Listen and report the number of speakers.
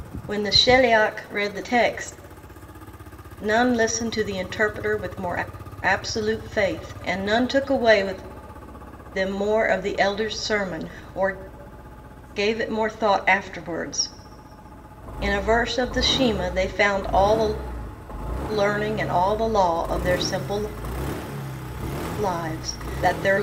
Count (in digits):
1